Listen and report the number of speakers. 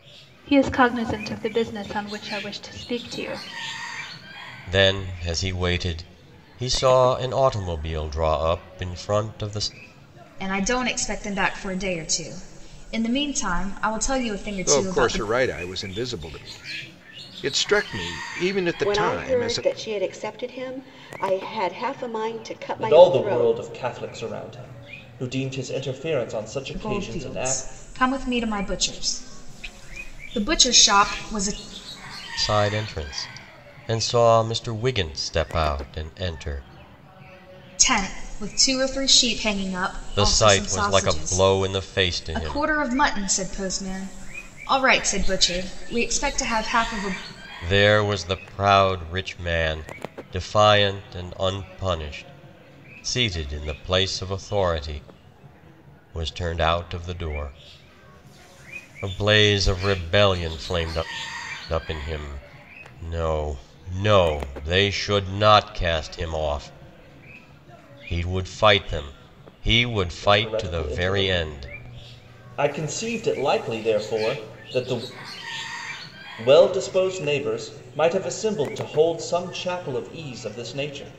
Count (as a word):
six